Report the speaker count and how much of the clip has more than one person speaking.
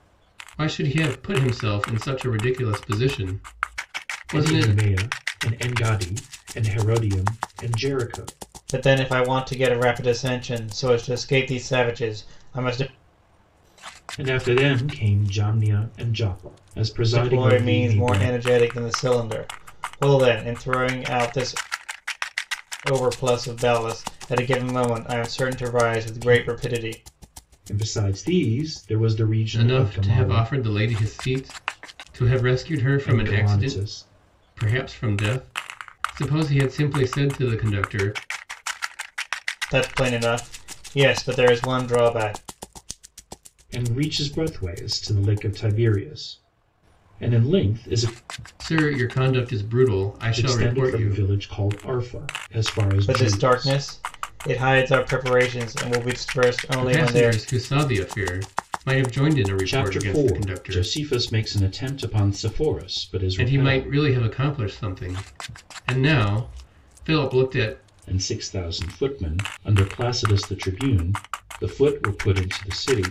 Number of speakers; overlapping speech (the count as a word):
three, about 12%